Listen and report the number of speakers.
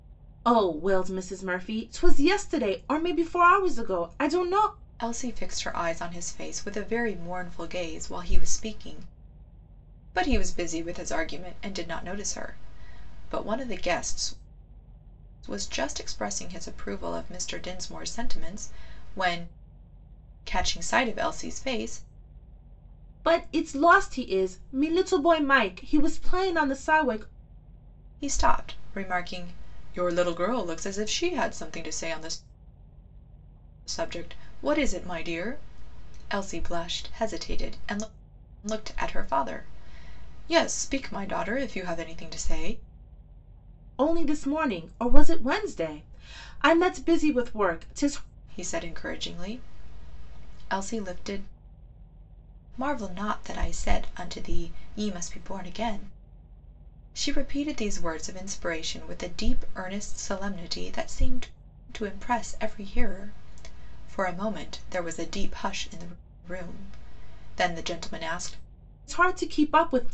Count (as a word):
two